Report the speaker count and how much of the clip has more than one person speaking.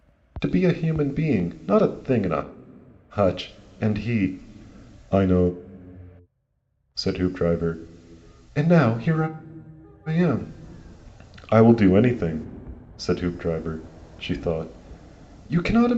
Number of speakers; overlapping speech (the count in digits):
1, no overlap